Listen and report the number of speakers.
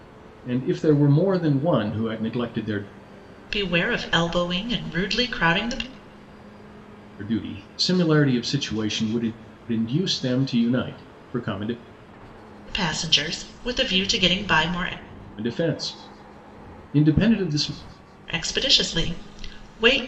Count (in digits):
2